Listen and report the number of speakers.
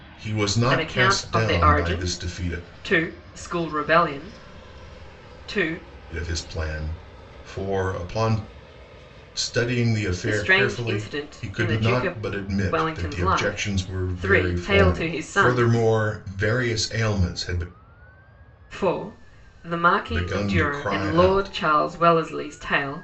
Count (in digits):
2